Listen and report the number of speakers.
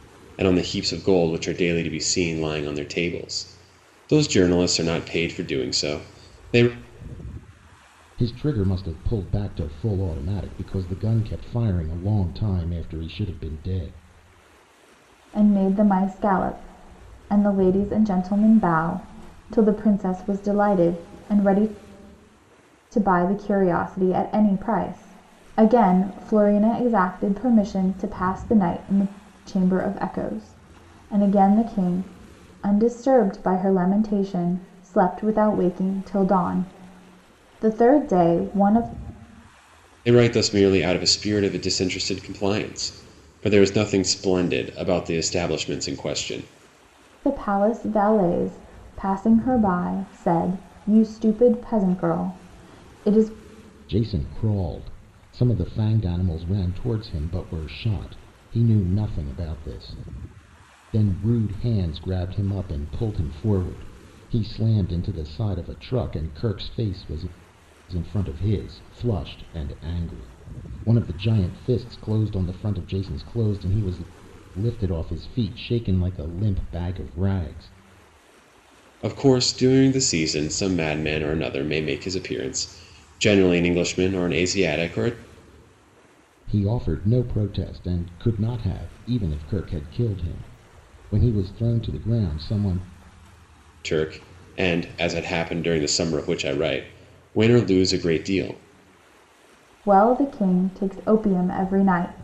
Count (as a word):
three